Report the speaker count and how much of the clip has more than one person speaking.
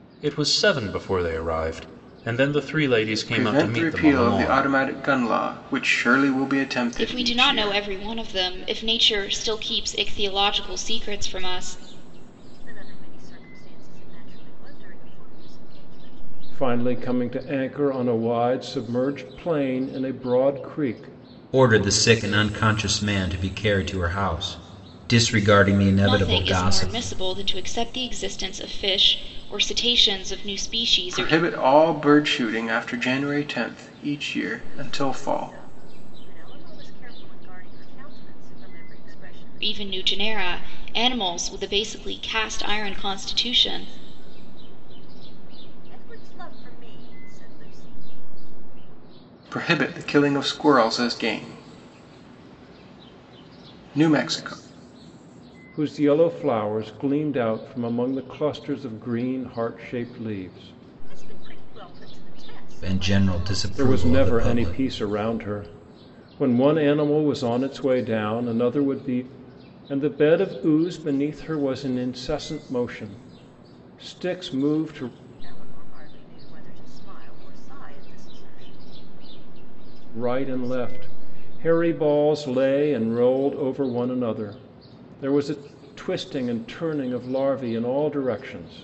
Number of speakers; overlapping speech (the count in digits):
6, about 10%